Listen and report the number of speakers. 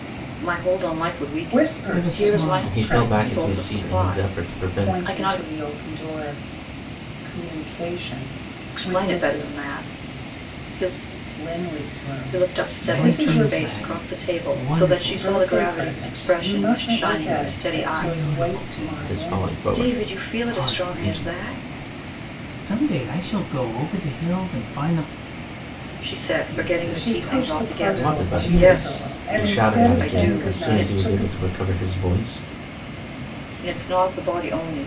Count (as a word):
four